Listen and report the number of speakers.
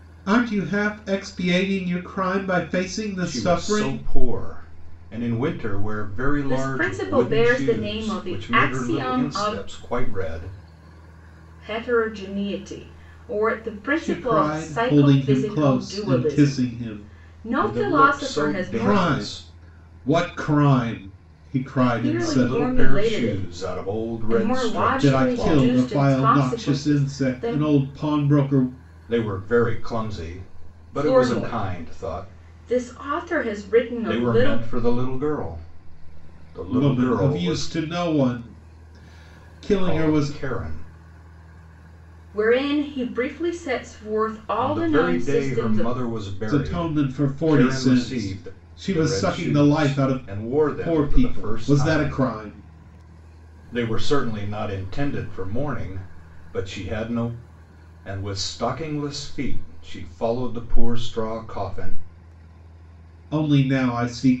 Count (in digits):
3